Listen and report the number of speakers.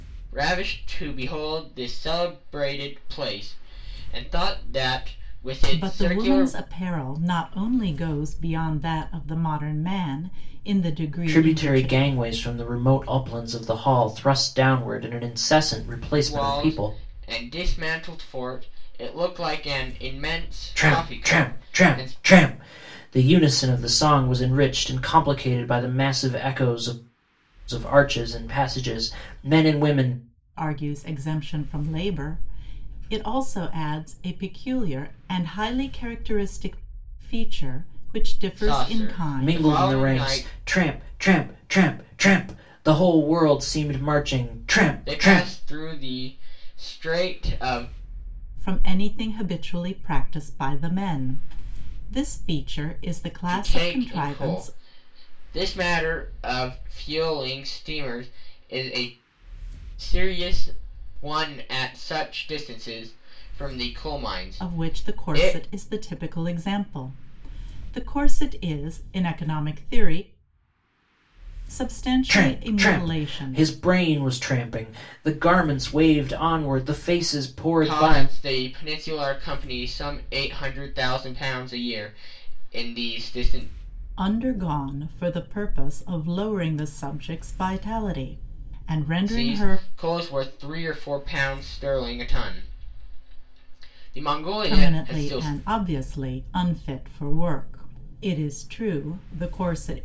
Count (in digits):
3